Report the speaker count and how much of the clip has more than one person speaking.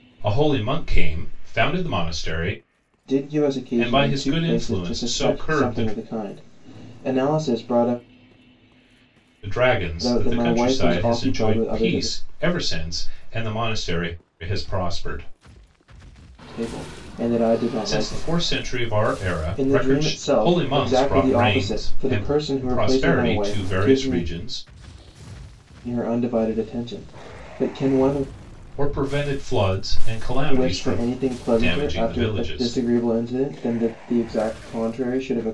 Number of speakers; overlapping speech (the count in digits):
2, about 30%